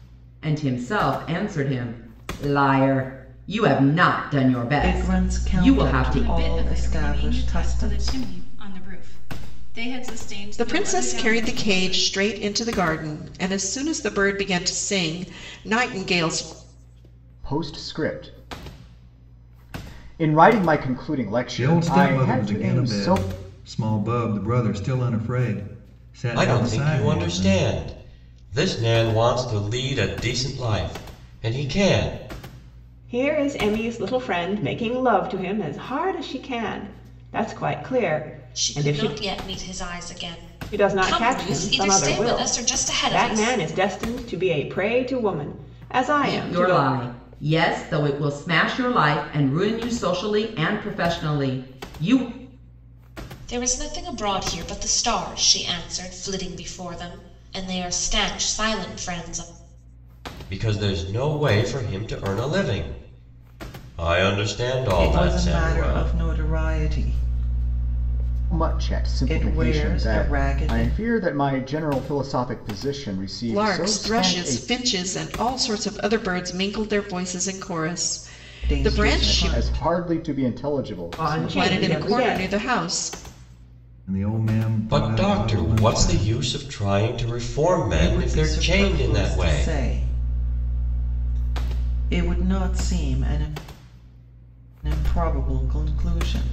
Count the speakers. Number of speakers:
nine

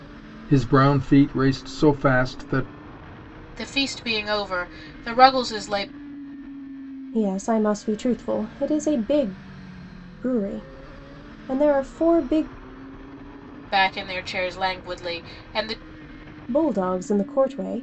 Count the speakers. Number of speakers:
three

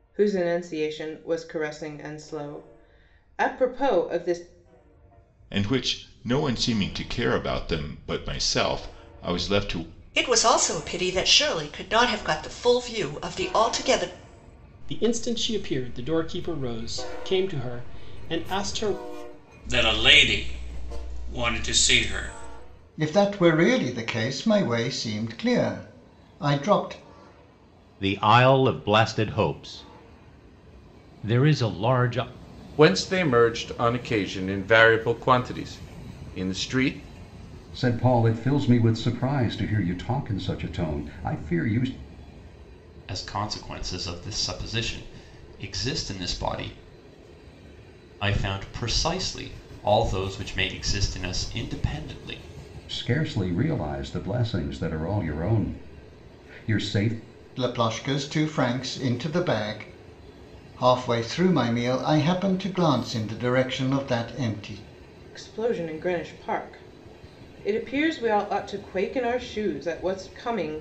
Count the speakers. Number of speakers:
ten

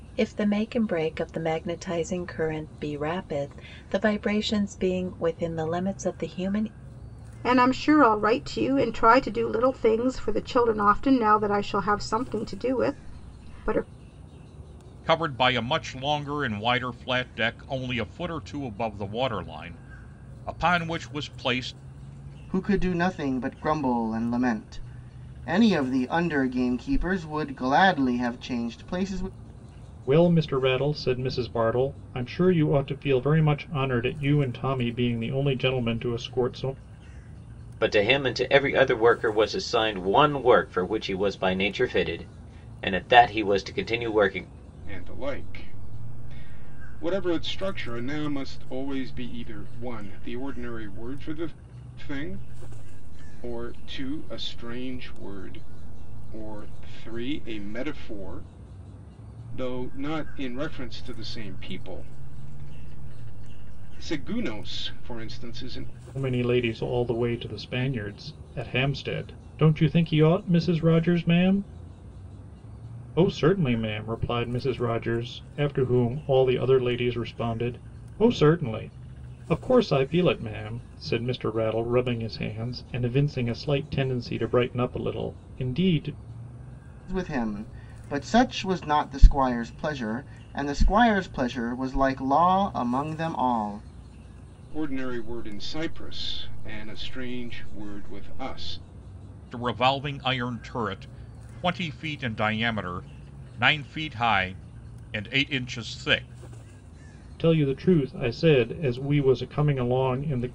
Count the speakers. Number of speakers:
seven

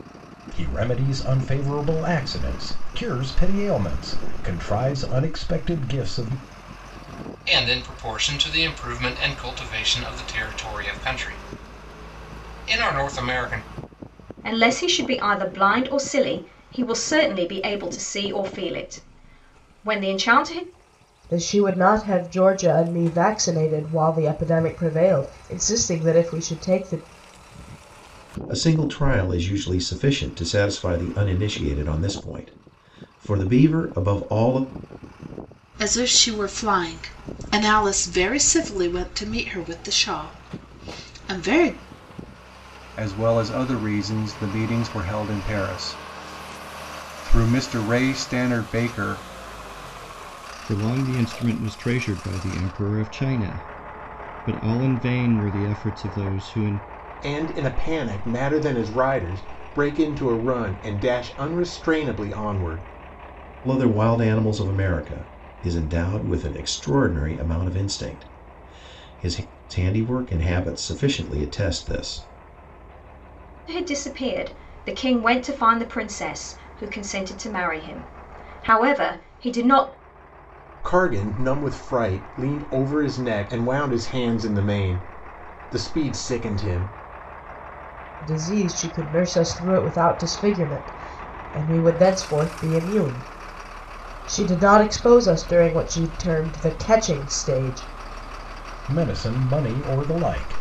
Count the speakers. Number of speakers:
nine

